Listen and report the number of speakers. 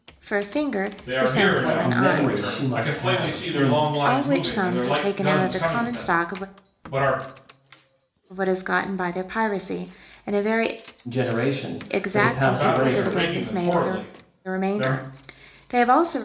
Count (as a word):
three